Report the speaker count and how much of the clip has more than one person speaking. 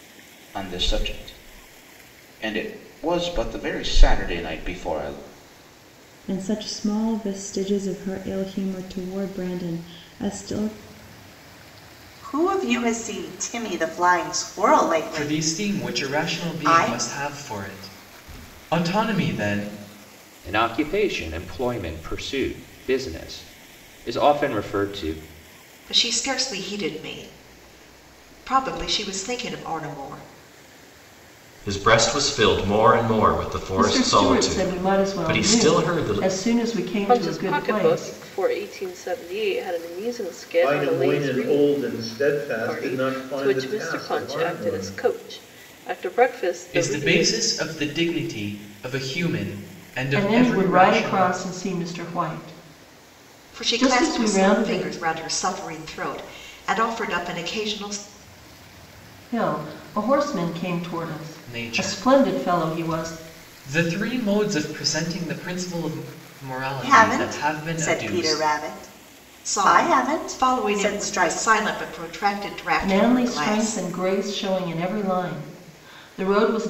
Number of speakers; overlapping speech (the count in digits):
10, about 25%